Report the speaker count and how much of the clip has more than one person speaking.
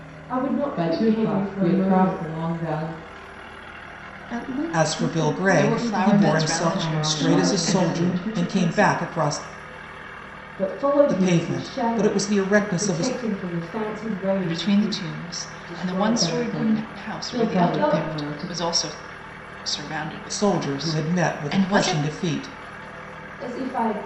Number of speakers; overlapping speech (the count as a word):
five, about 55%